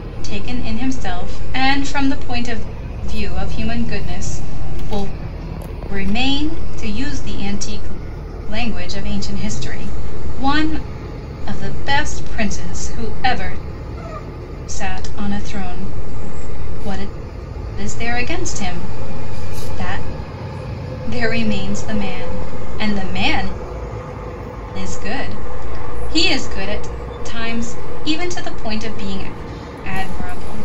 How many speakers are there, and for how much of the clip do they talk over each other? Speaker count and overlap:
one, no overlap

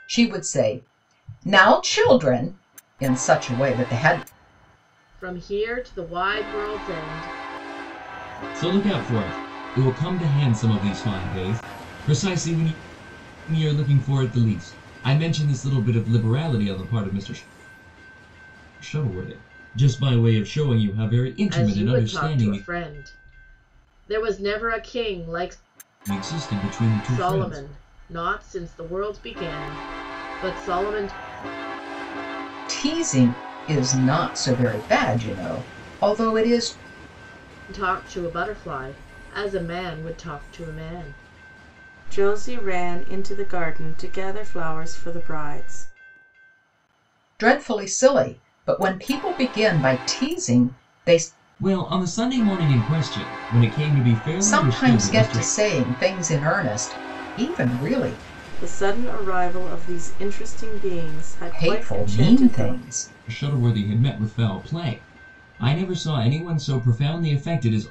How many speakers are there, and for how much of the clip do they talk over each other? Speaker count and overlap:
three, about 6%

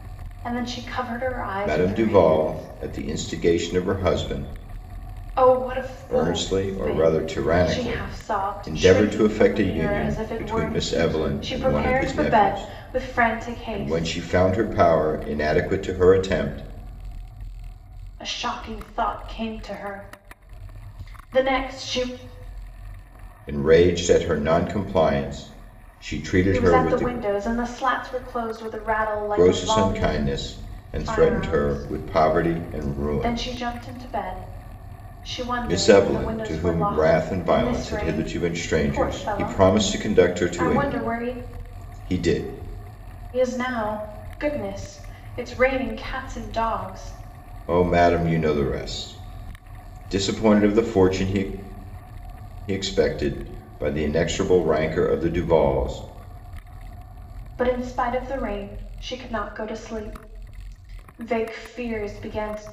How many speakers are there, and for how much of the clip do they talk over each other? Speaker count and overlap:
two, about 31%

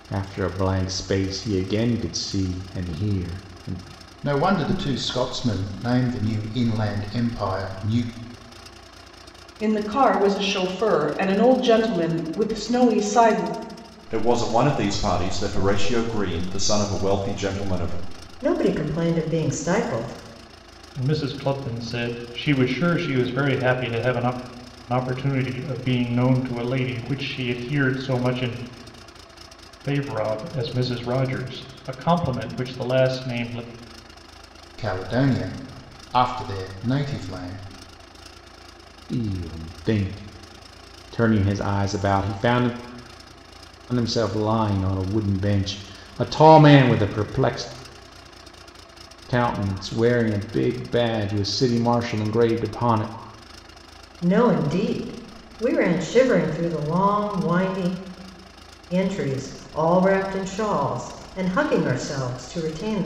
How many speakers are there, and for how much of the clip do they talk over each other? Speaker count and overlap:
six, no overlap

